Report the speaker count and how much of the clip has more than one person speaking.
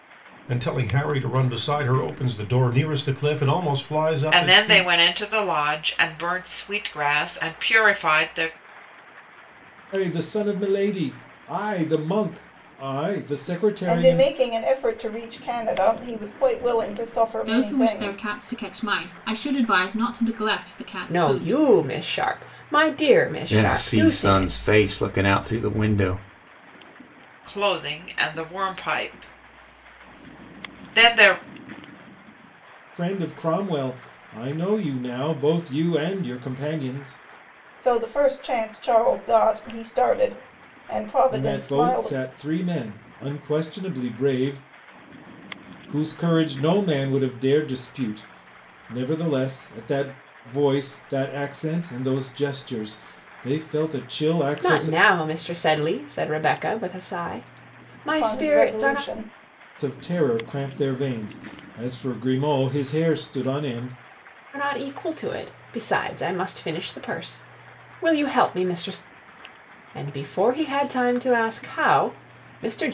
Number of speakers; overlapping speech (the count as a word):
seven, about 8%